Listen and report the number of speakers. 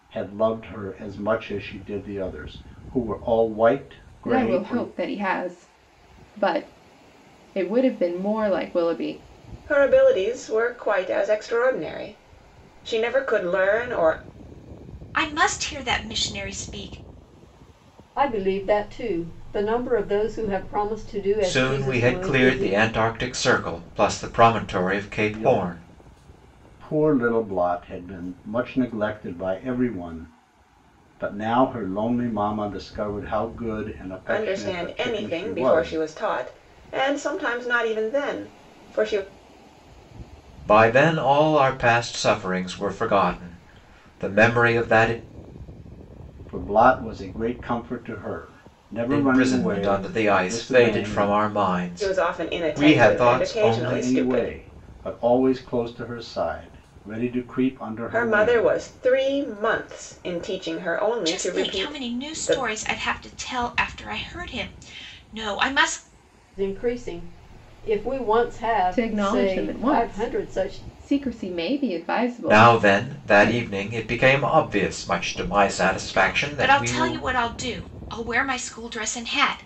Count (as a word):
six